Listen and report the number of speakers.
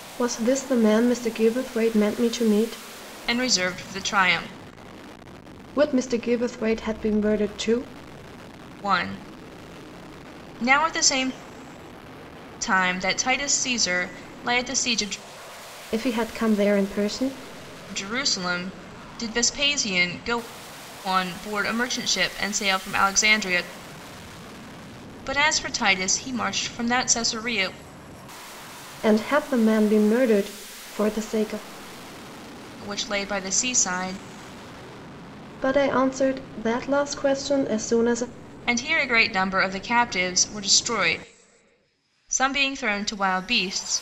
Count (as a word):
two